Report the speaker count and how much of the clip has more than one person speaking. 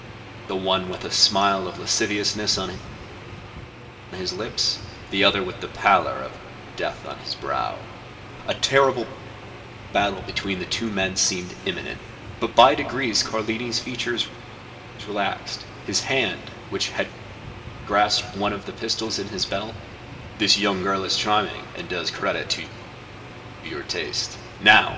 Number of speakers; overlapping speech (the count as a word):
one, no overlap